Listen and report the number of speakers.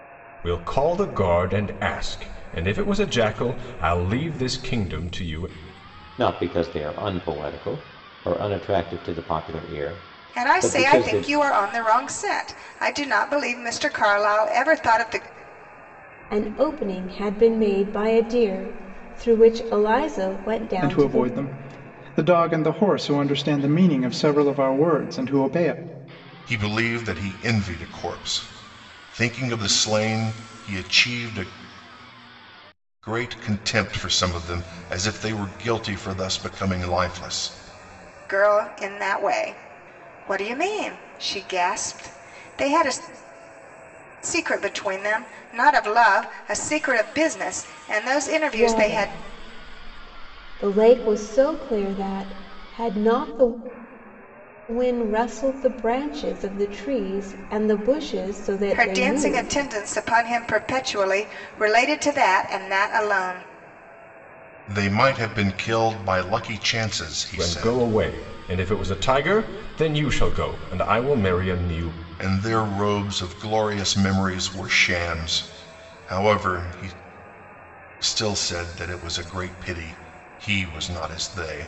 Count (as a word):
six